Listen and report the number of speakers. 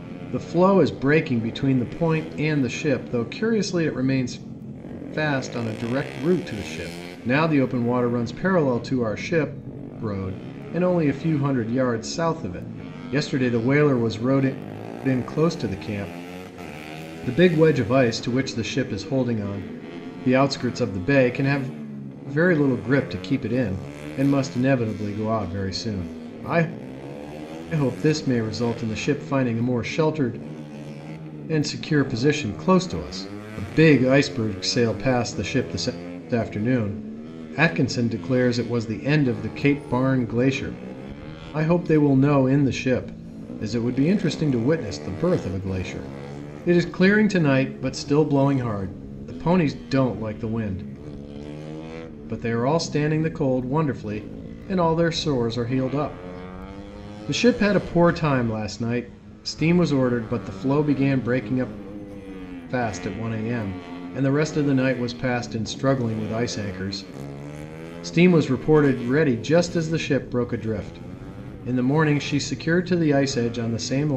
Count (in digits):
1